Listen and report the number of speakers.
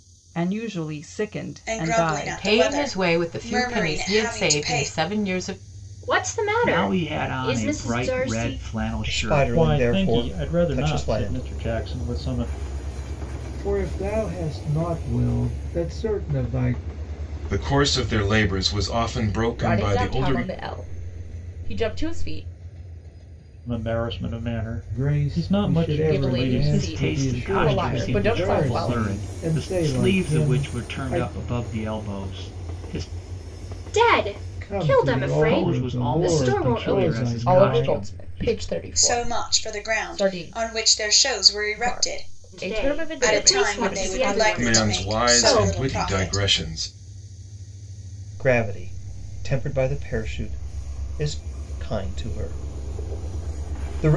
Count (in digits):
10